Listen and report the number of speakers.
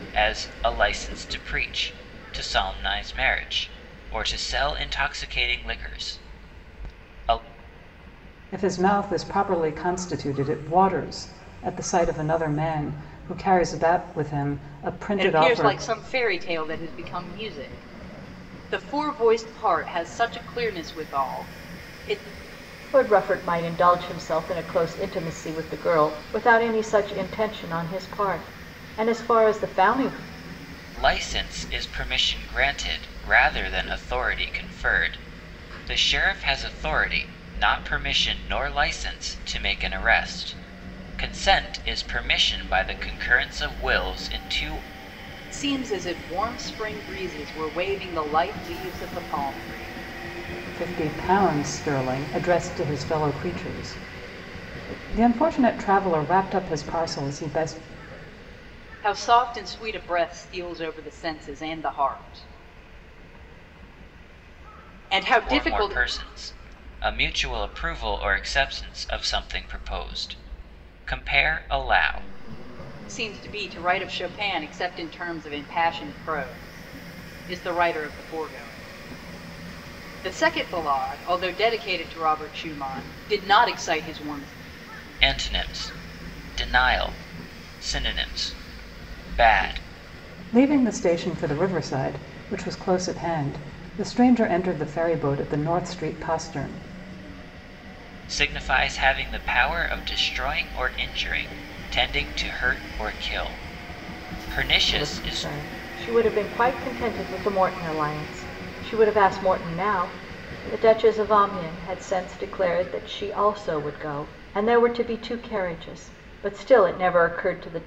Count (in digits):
4